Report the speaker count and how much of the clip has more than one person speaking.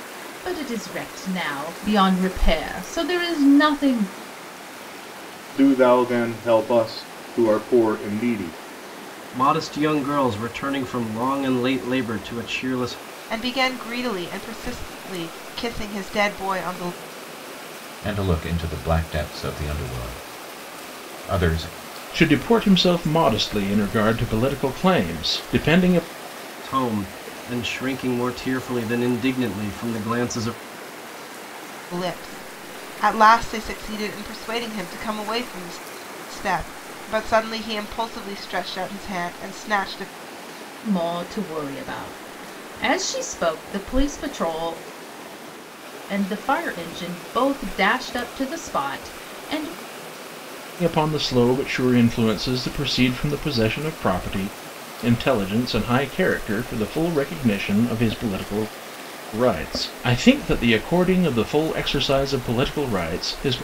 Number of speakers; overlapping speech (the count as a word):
six, no overlap